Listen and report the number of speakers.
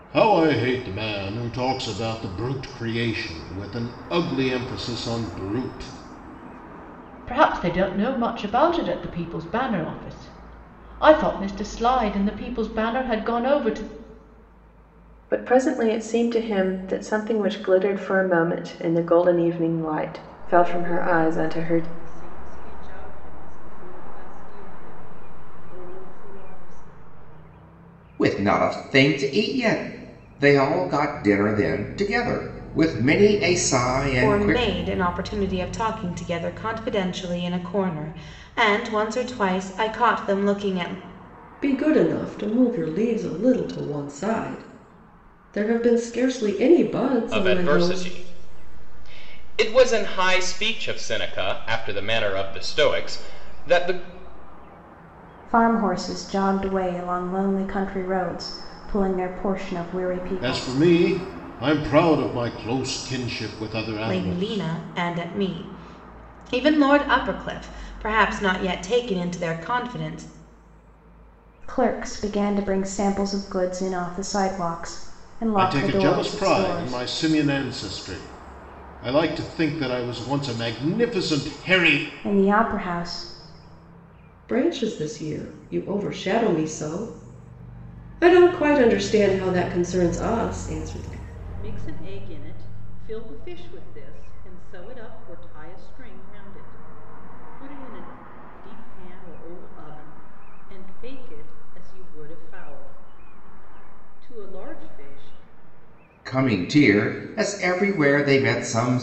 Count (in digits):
9